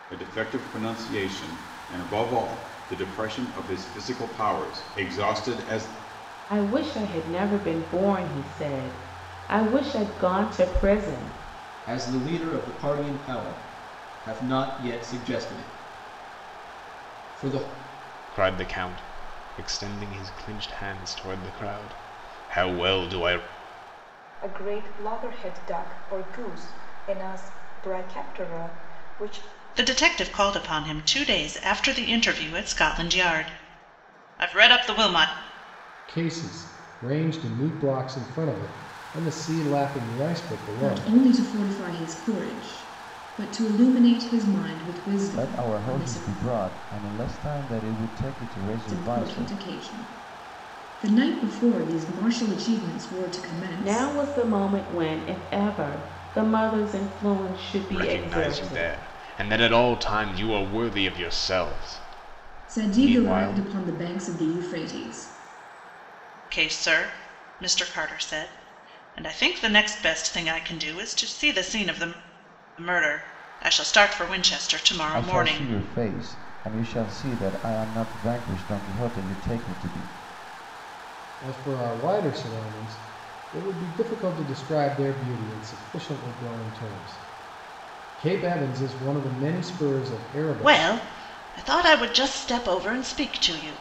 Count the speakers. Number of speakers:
9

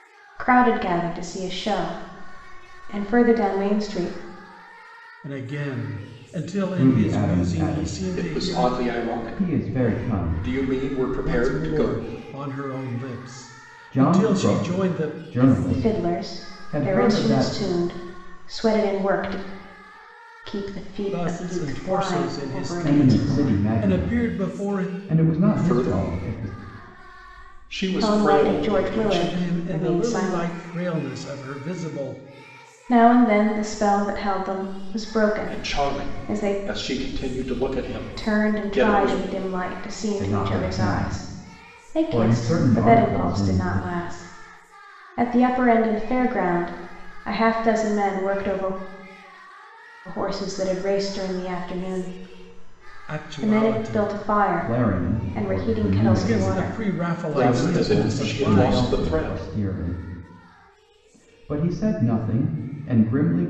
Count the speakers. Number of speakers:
4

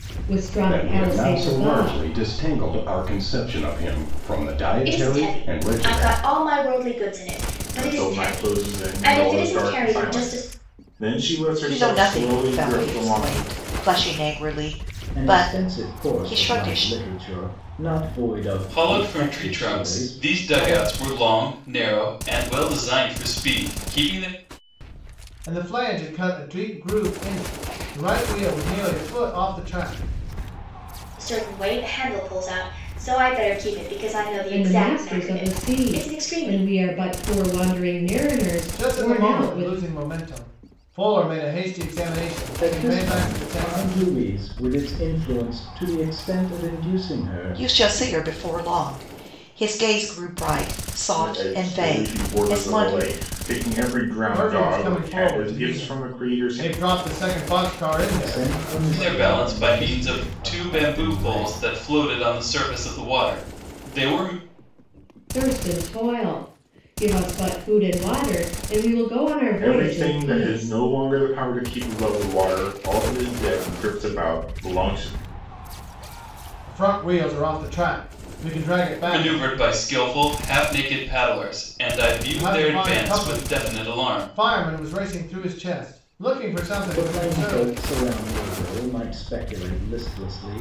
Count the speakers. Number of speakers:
8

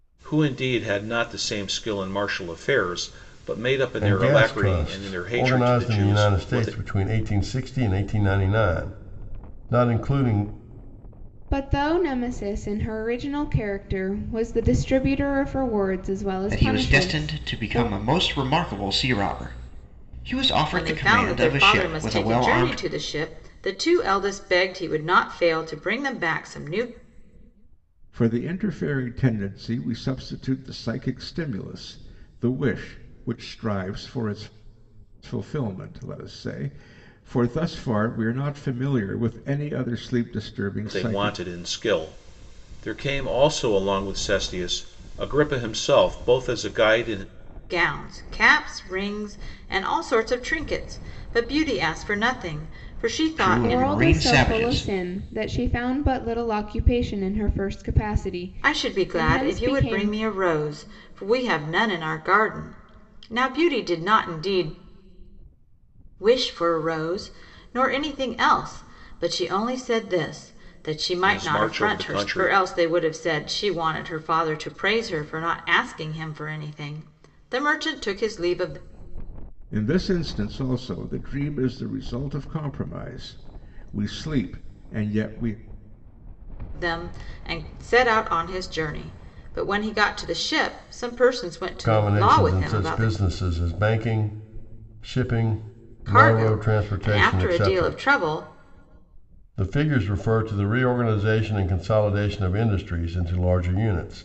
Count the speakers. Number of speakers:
6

